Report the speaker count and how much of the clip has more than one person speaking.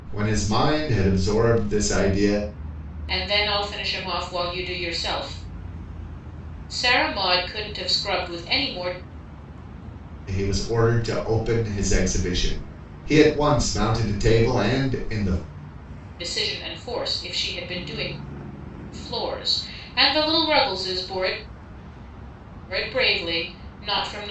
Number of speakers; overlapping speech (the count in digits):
2, no overlap